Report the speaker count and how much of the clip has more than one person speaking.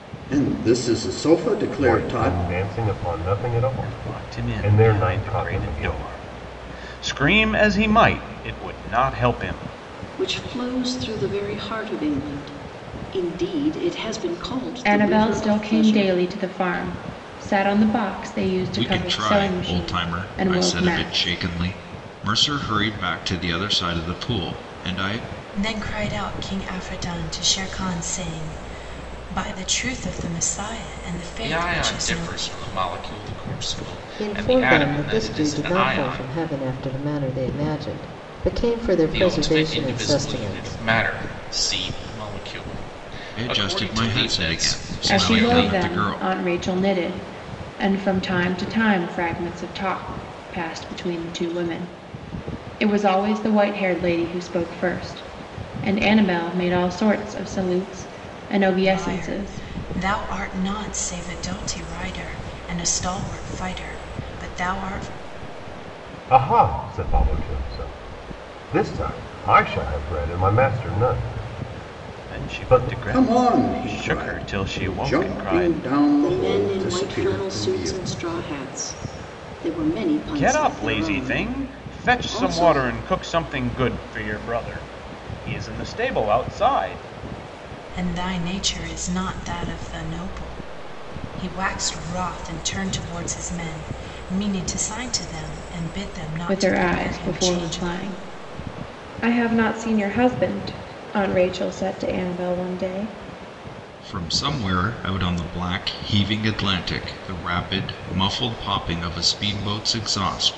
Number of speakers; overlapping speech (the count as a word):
nine, about 23%